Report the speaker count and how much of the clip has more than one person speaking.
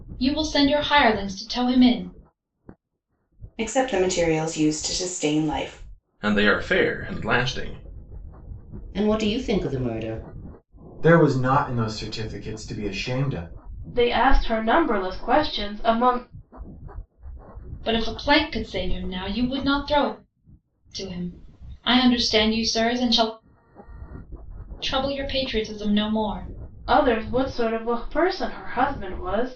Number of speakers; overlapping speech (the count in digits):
6, no overlap